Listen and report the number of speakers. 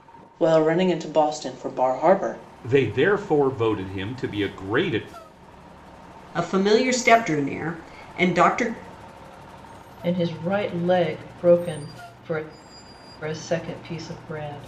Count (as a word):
four